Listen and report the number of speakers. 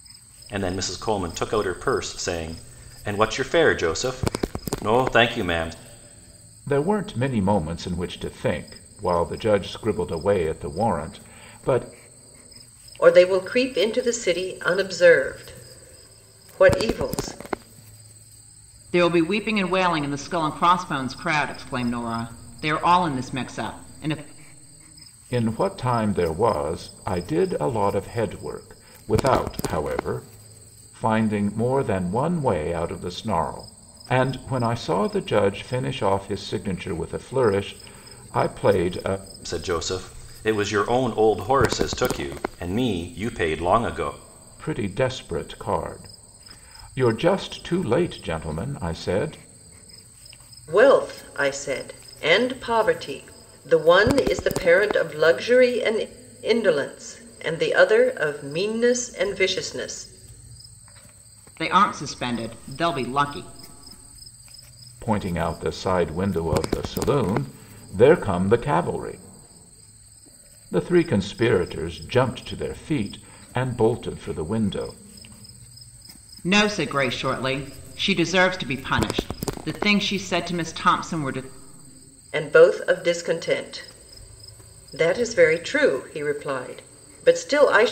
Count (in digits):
4